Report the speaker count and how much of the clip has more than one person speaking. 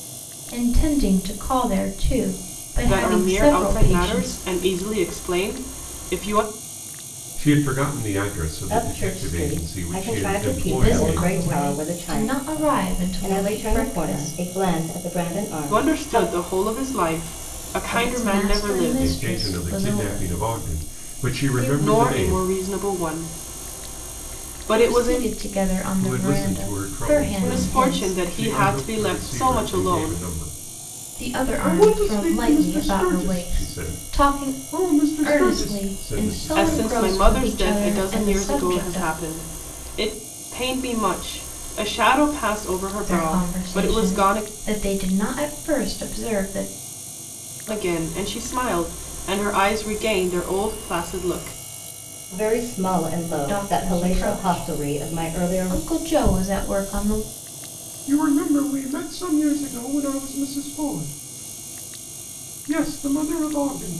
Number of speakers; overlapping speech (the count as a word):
four, about 45%